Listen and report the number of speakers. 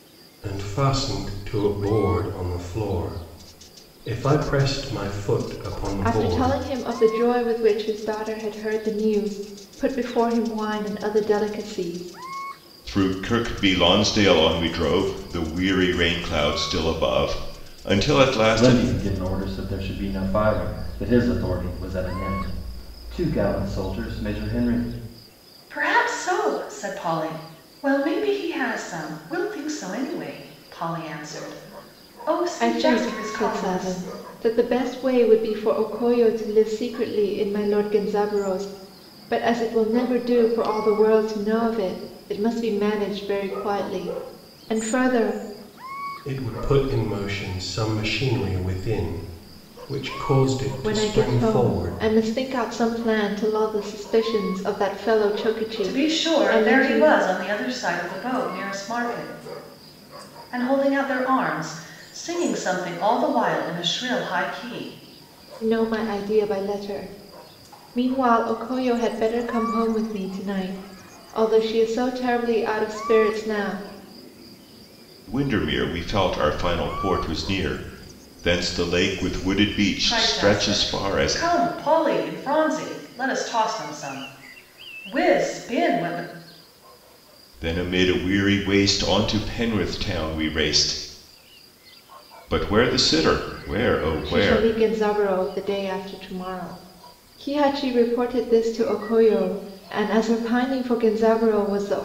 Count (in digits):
5